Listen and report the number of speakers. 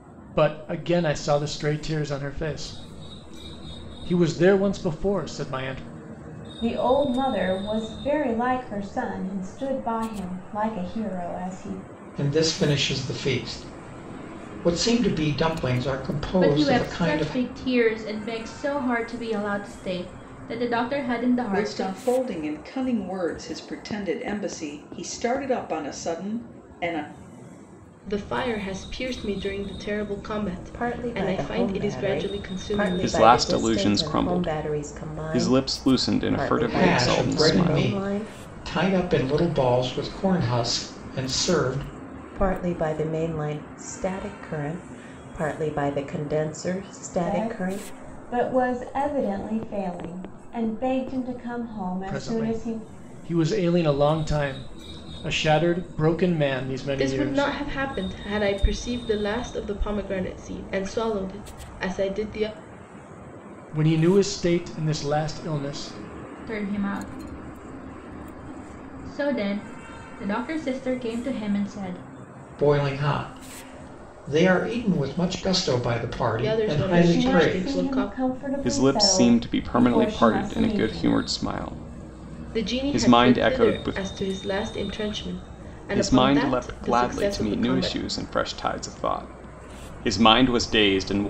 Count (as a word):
eight